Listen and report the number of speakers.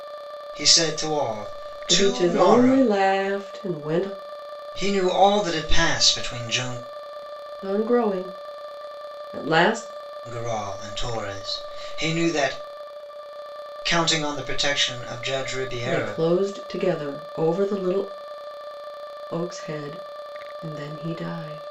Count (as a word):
two